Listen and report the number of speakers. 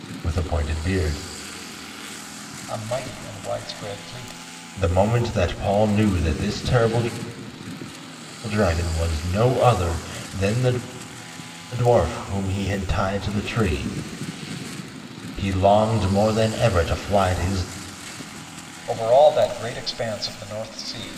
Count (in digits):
2